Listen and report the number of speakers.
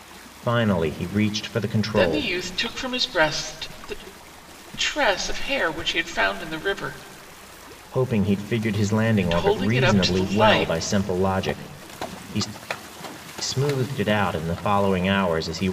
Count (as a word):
two